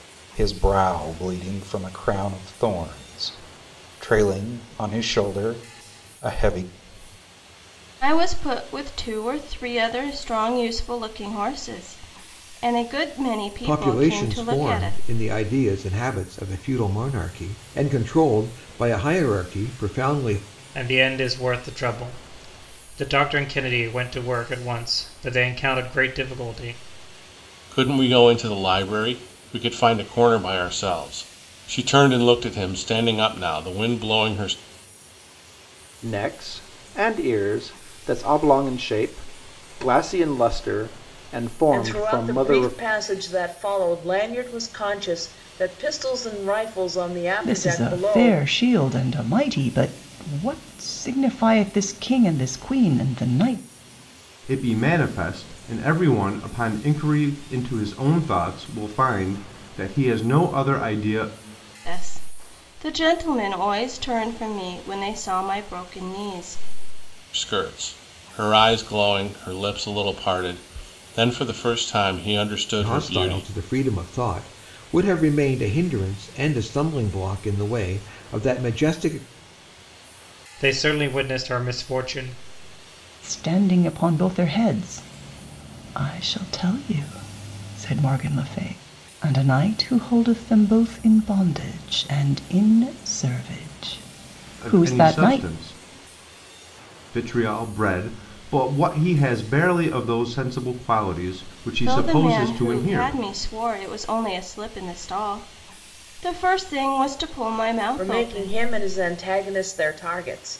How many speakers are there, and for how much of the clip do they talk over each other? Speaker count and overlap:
nine, about 7%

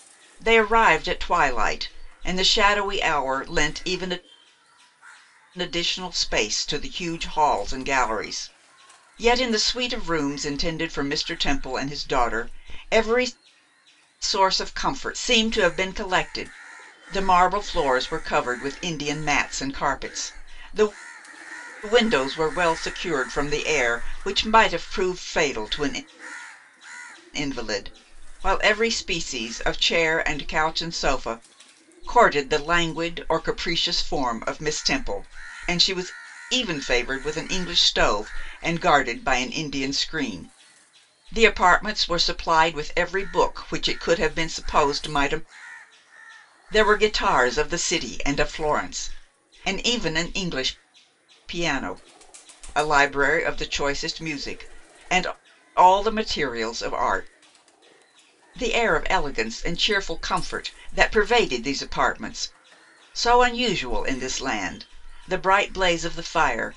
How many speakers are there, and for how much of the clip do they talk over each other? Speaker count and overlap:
one, no overlap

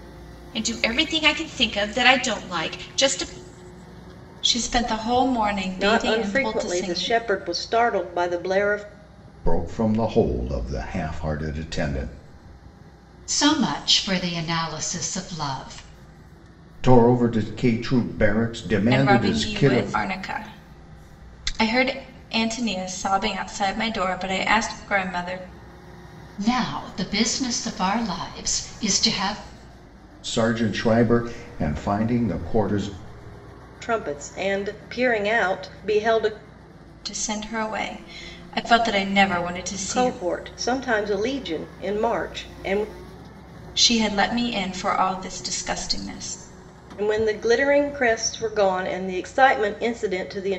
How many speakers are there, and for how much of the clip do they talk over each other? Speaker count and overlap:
five, about 6%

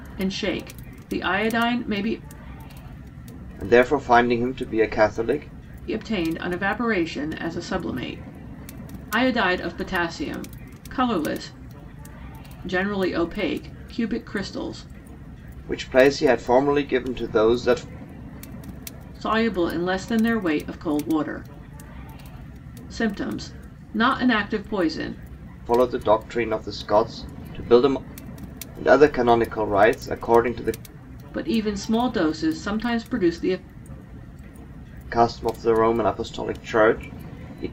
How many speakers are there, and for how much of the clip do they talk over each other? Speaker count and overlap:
two, no overlap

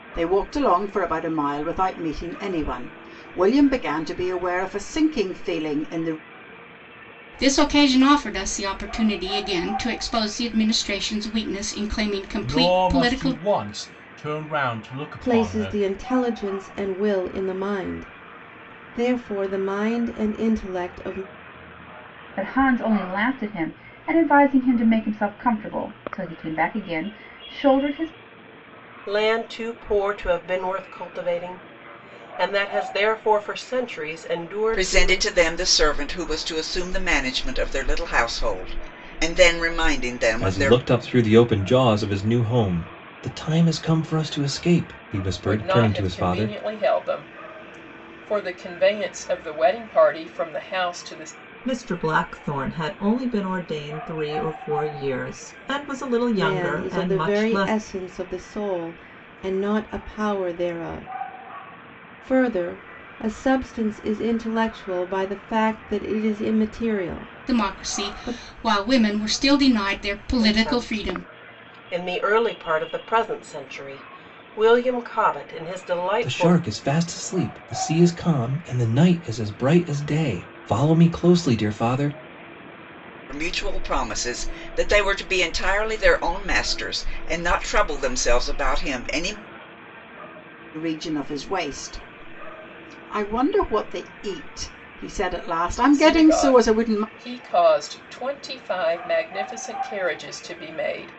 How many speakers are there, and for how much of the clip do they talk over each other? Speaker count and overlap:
ten, about 9%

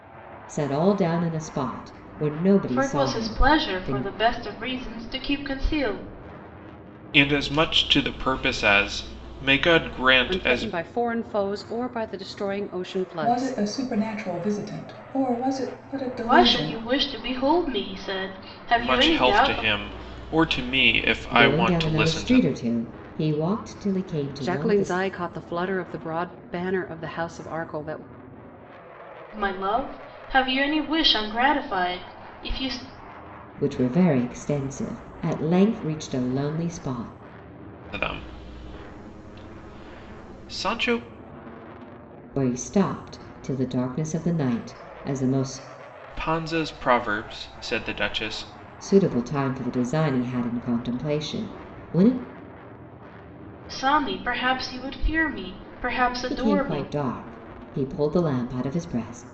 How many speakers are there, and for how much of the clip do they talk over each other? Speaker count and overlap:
five, about 11%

